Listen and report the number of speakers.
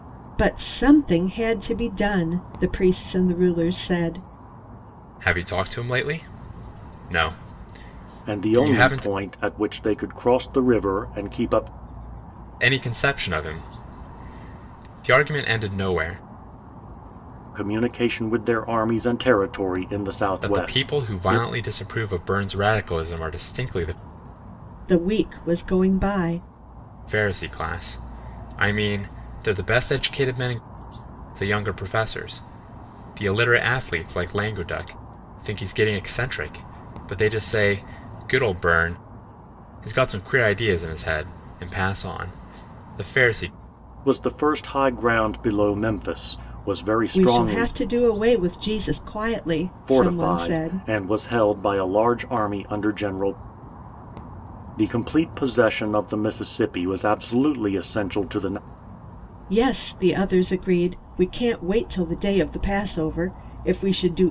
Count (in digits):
3